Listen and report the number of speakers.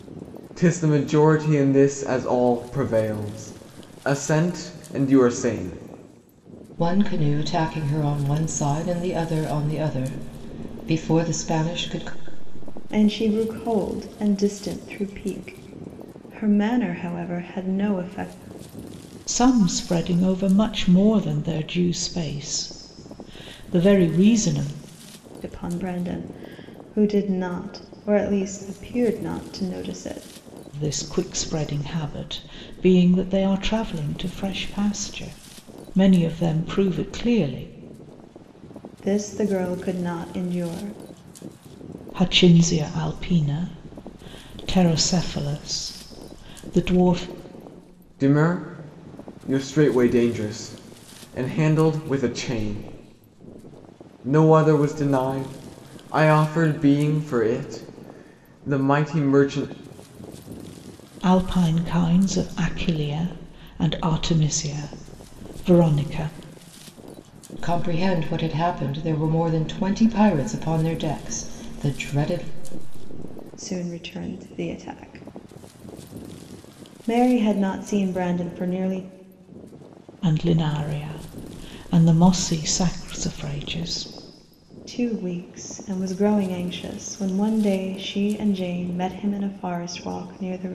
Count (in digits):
4